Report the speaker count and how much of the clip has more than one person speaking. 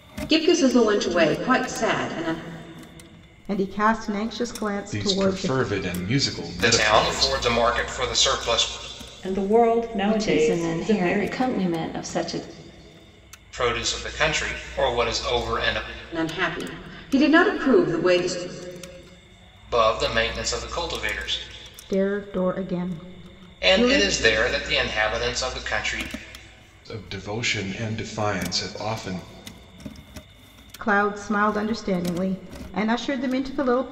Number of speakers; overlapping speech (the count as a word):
six, about 10%